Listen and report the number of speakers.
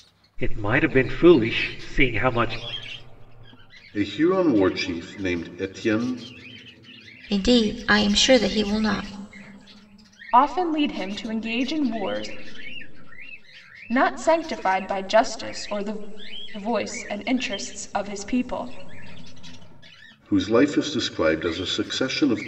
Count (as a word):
four